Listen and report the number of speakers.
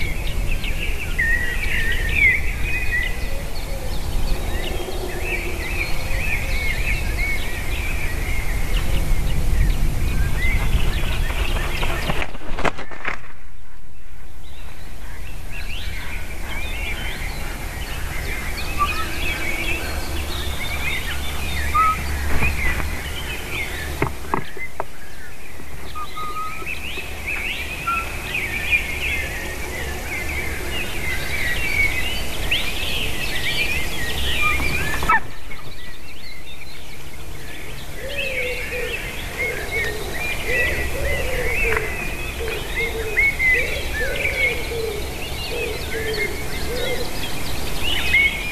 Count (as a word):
zero